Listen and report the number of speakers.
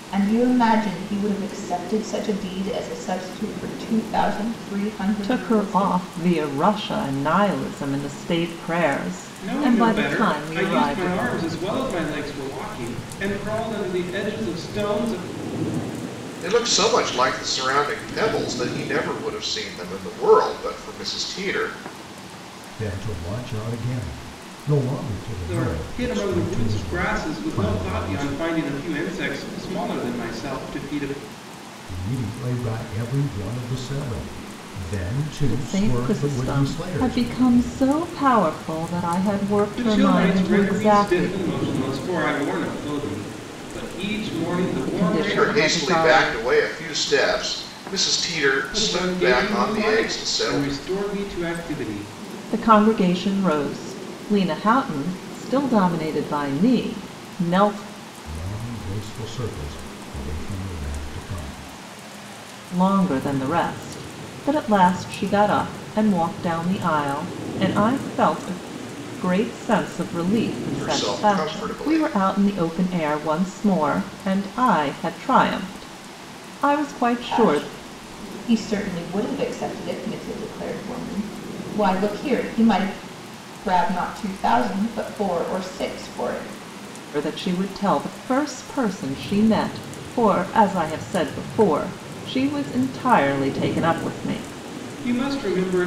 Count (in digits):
5